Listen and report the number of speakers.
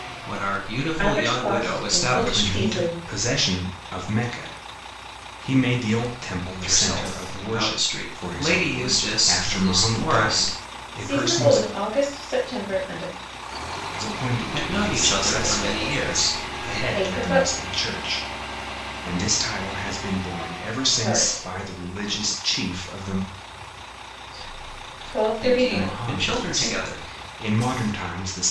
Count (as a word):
three